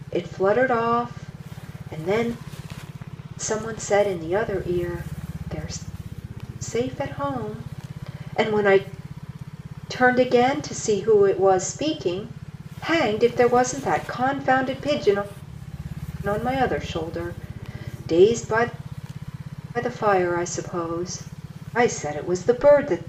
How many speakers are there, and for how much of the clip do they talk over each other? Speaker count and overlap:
one, no overlap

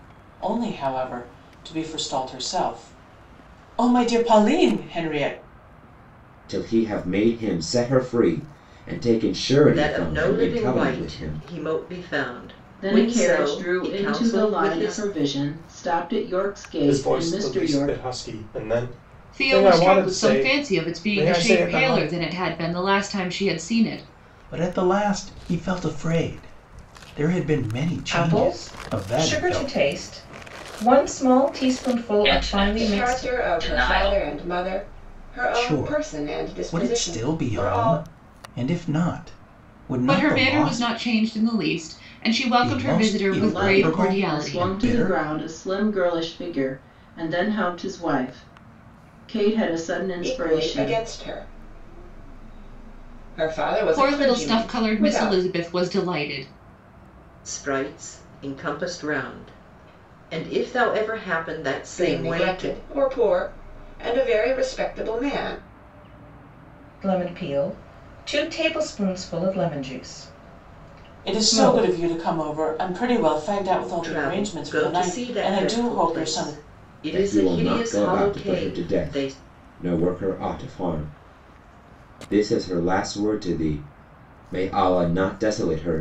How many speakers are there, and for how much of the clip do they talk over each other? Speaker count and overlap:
ten, about 31%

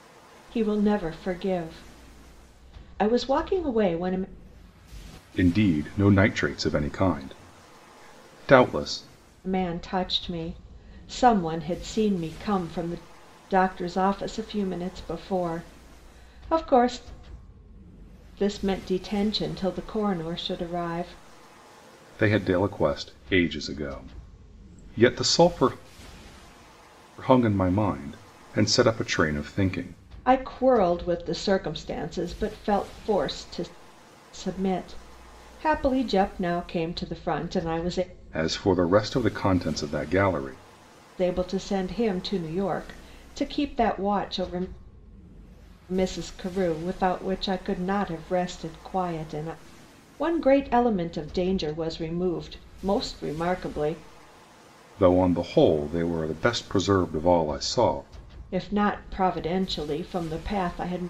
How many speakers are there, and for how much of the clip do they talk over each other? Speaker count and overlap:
two, no overlap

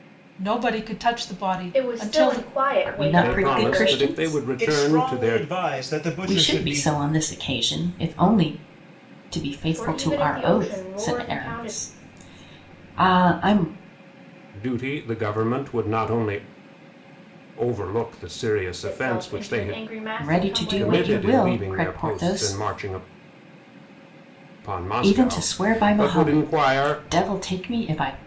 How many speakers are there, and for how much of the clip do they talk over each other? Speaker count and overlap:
five, about 41%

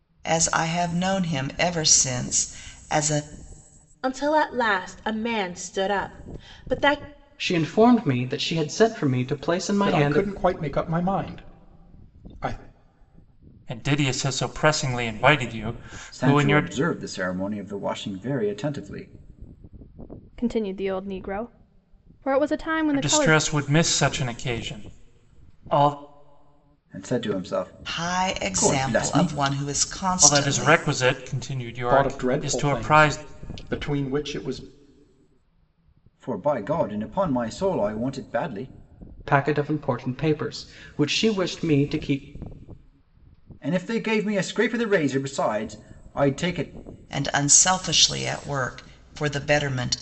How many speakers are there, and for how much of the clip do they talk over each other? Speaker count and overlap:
seven, about 10%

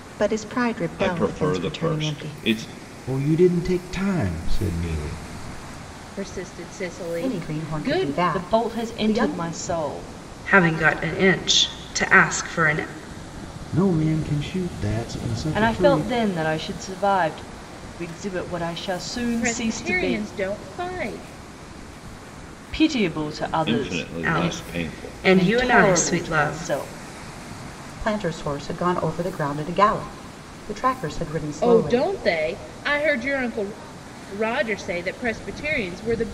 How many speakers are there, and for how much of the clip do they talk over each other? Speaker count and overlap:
seven, about 23%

